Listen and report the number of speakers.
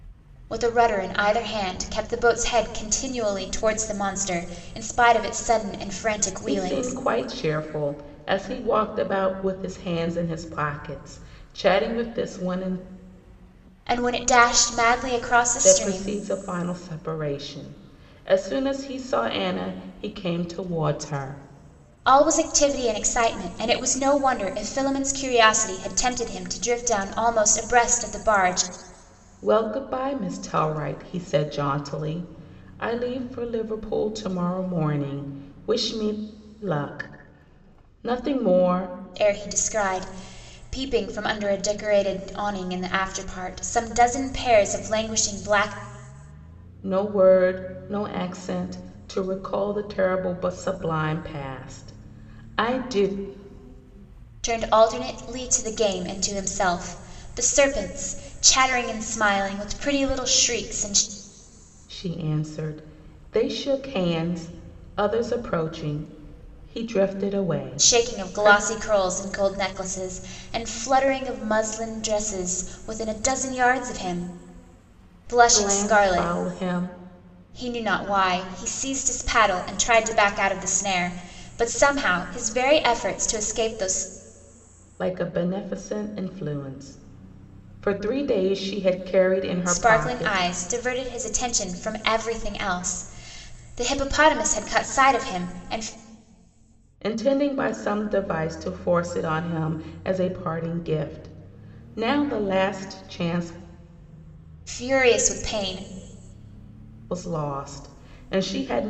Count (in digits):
2